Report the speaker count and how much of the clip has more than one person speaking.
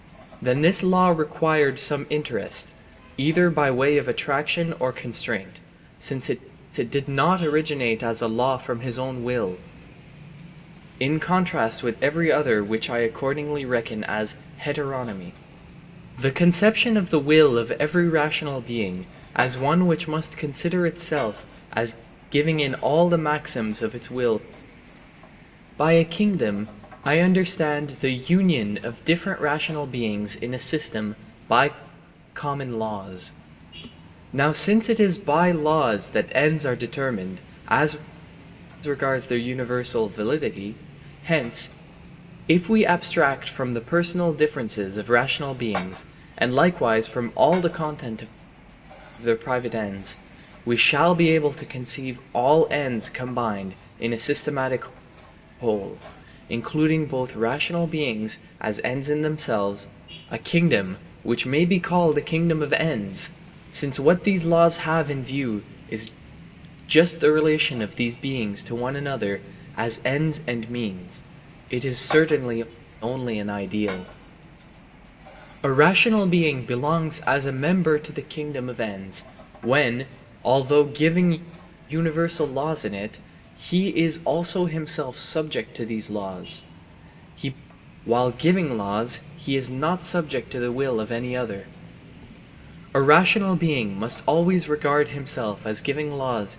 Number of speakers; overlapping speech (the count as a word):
one, no overlap